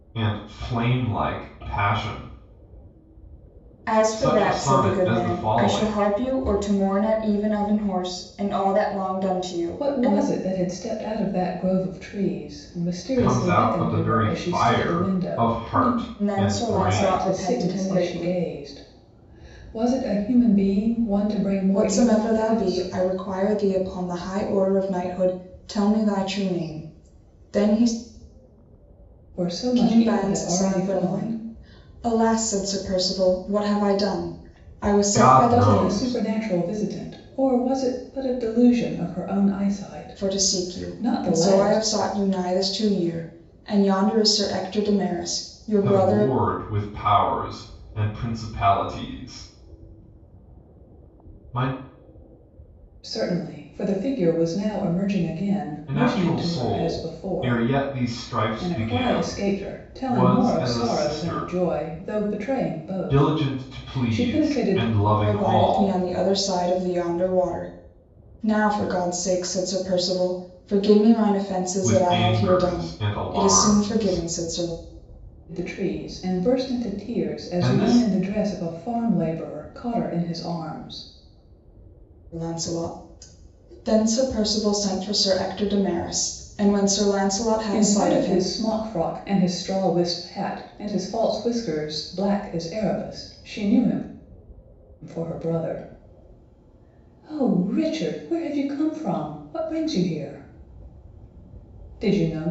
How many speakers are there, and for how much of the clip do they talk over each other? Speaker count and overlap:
3, about 27%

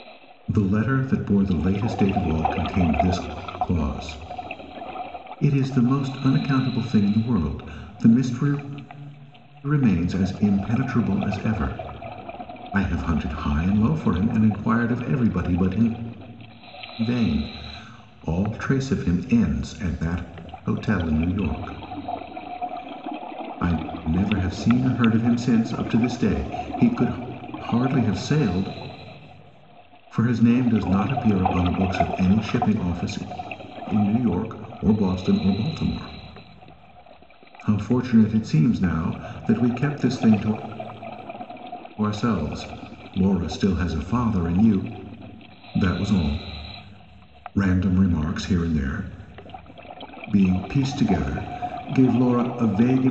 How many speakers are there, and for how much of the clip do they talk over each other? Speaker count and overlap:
1, no overlap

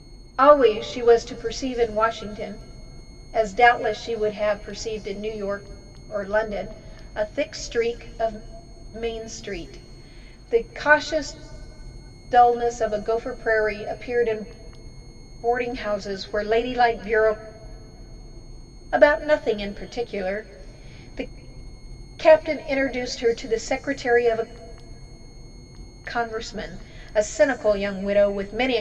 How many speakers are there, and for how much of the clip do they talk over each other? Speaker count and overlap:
1, no overlap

